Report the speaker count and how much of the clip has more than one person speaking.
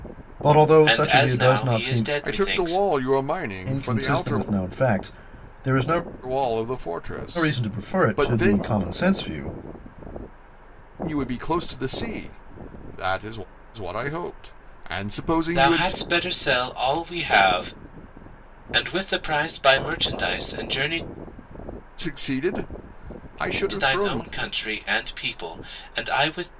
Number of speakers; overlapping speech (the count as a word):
three, about 19%